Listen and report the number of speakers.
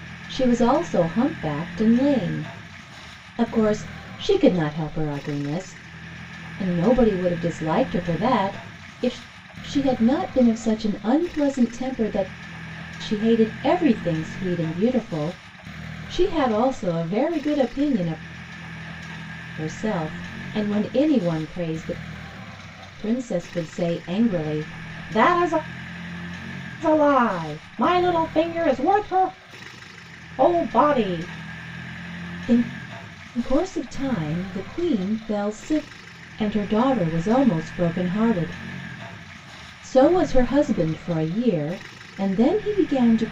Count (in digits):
1